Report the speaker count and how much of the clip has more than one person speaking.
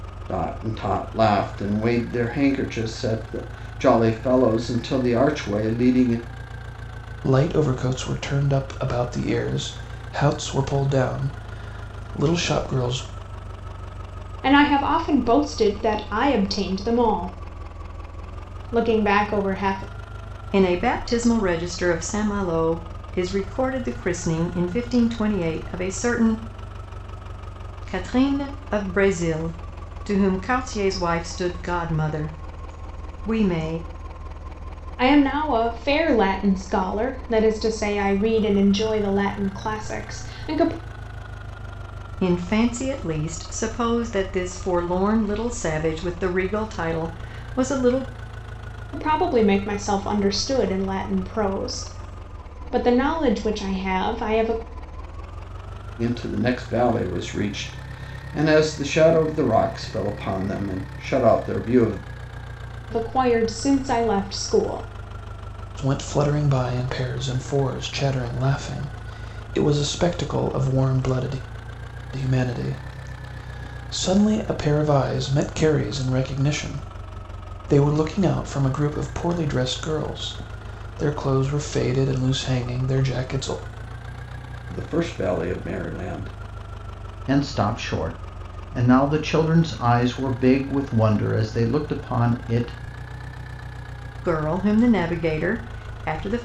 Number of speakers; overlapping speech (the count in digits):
4, no overlap